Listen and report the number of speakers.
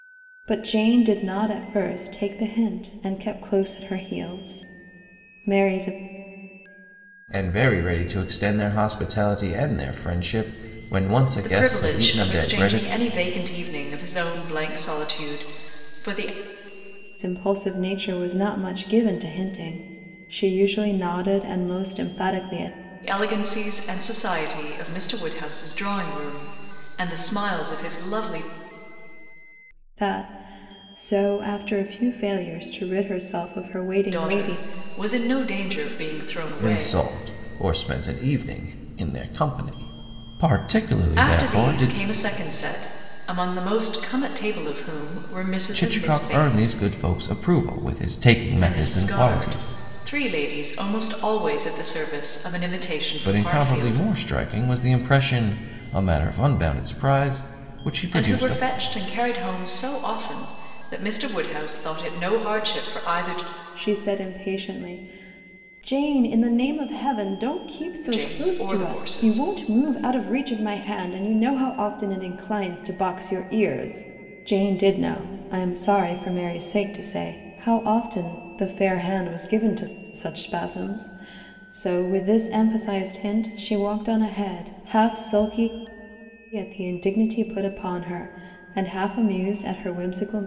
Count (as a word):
three